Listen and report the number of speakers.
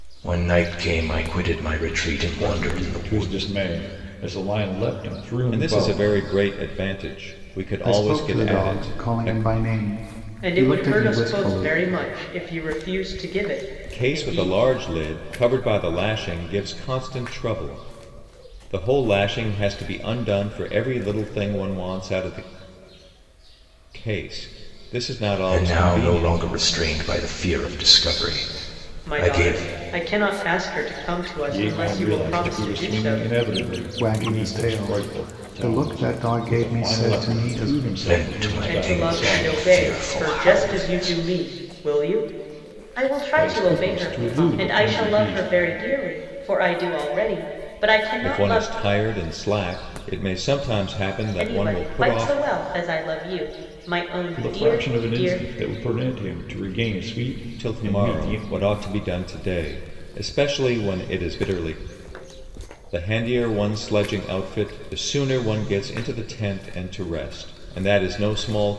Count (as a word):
five